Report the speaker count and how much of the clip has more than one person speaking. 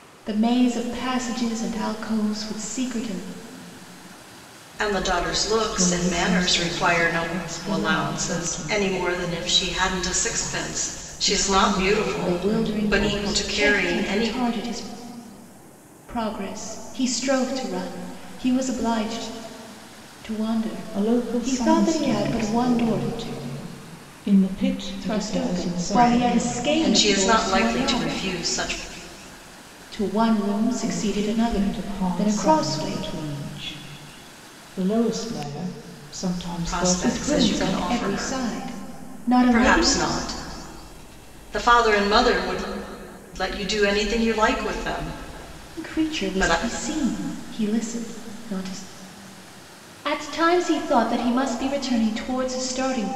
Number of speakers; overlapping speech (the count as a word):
three, about 33%